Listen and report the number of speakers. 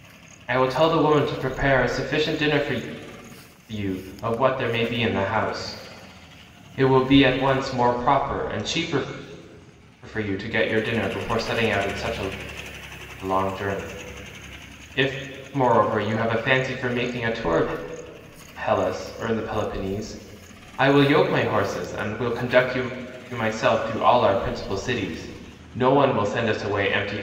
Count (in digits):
1